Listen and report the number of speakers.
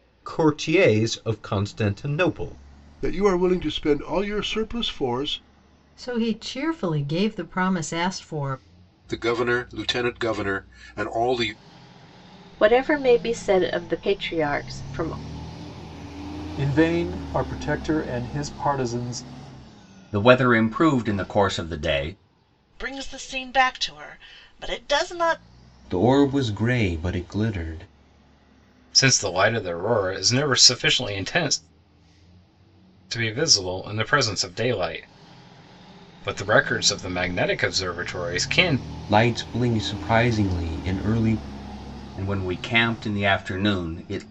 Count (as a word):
ten